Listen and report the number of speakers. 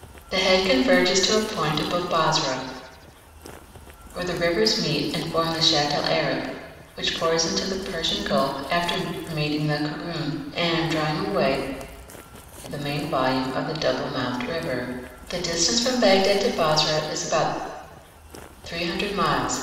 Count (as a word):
one